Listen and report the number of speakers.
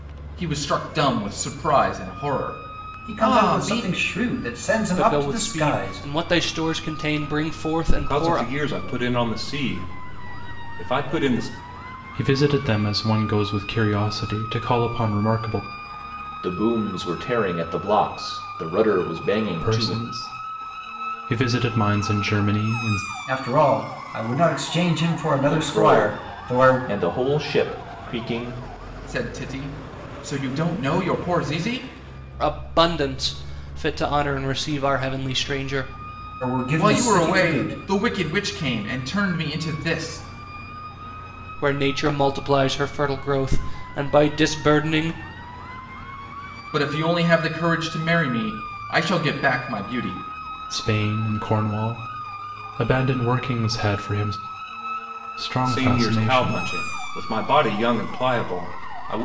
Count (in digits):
6